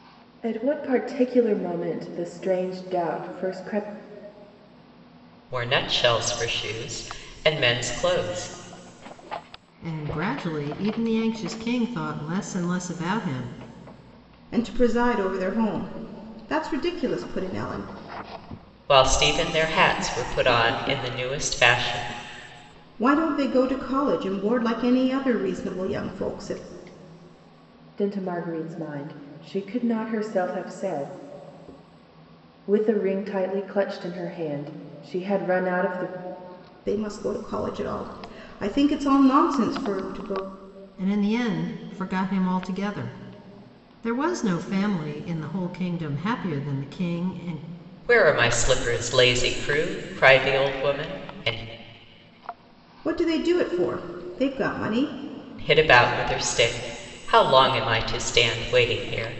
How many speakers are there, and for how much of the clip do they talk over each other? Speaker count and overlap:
4, no overlap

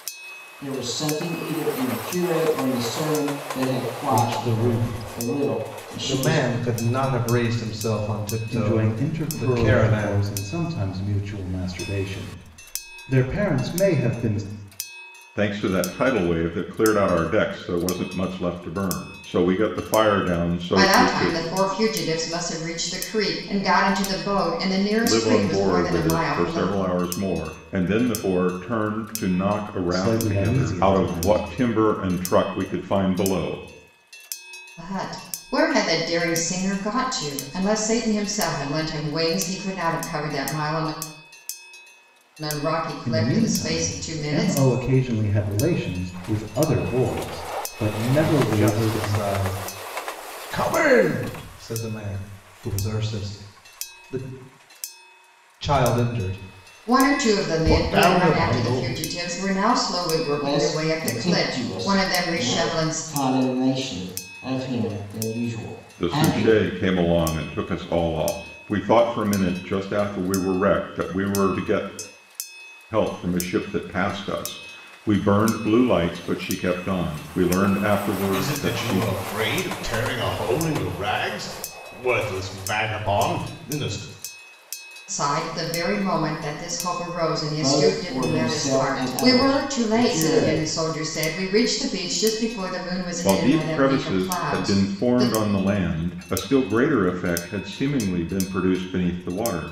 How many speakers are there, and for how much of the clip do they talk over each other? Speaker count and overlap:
5, about 22%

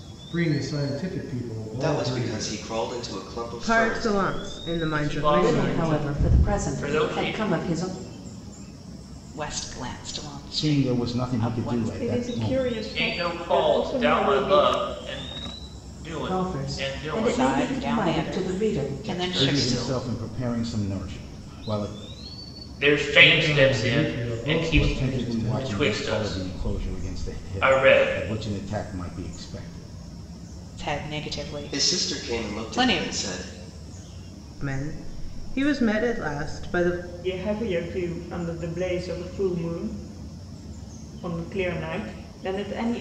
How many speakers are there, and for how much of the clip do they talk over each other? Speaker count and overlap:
8, about 42%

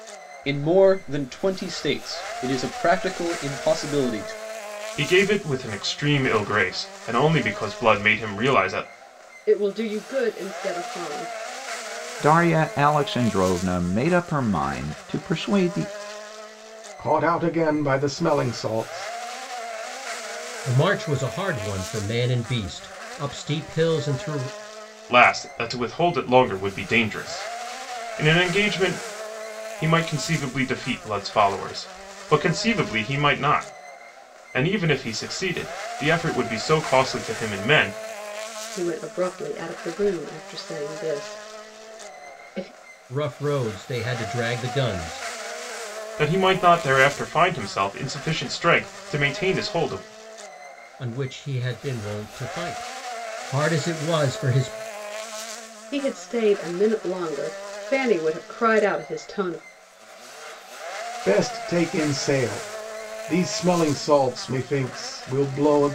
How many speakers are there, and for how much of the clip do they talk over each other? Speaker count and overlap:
6, no overlap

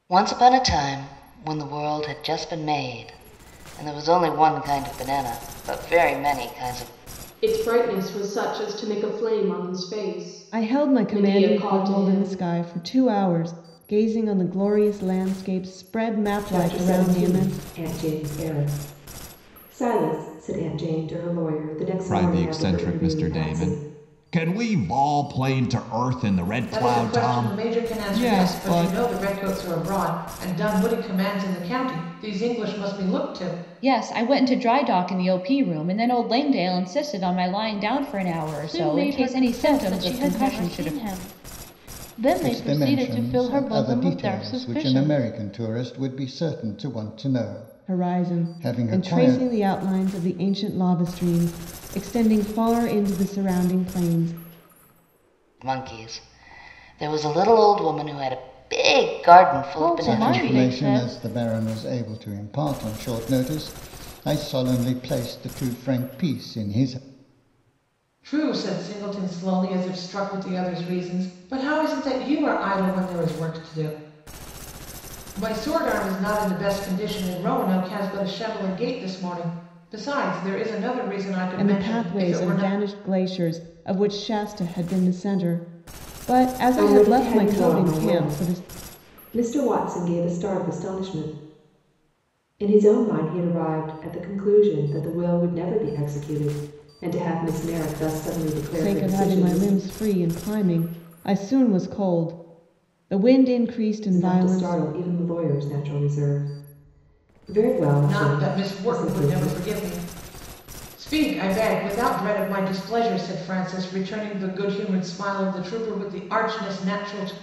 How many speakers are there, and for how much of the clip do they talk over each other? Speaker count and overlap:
9, about 19%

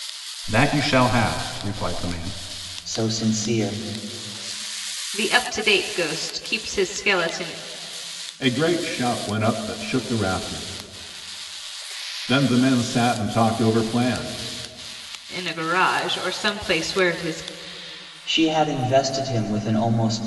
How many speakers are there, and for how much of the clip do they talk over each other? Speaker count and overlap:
4, no overlap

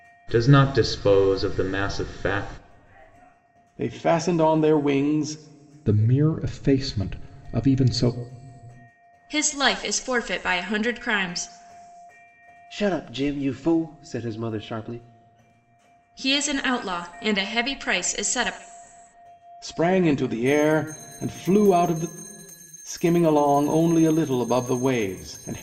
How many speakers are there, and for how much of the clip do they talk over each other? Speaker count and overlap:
5, no overlap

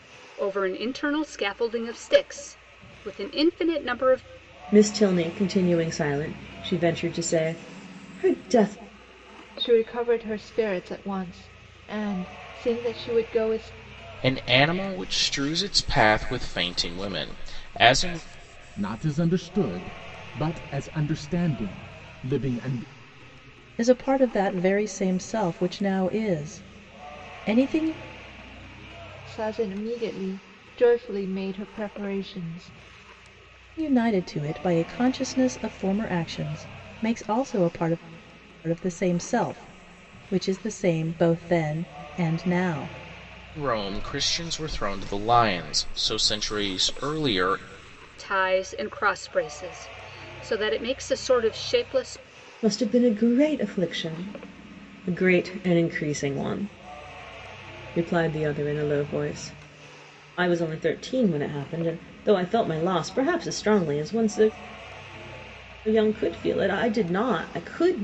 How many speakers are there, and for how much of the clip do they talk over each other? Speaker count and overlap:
6, no overlap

